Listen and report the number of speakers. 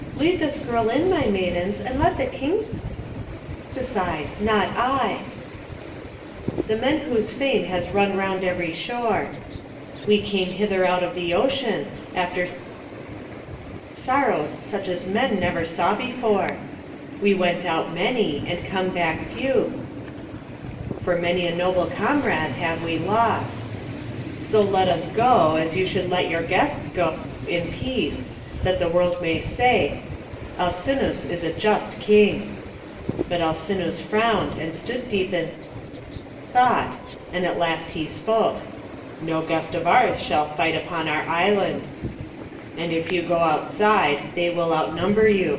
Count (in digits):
1